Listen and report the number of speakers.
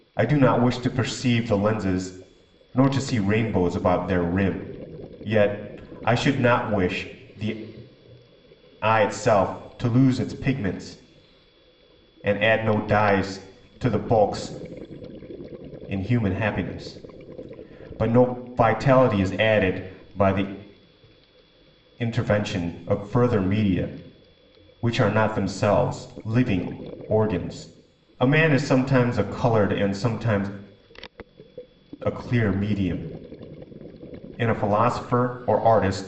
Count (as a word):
one